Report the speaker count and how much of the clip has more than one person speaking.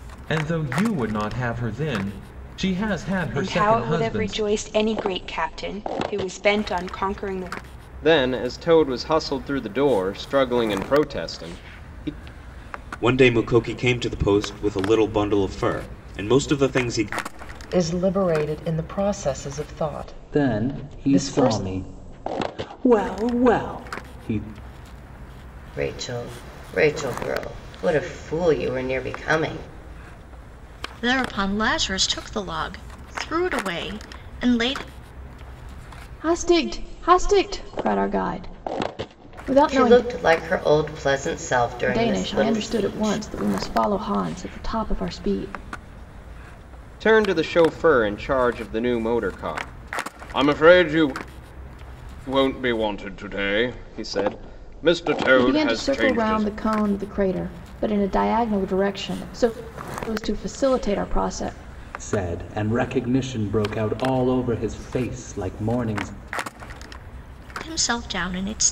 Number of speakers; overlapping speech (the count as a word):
nine, about 8%